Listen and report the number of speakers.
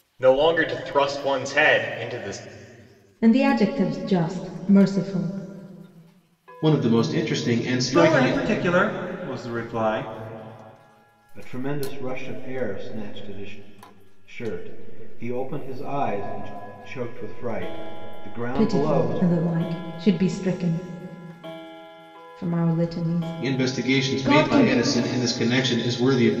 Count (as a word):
five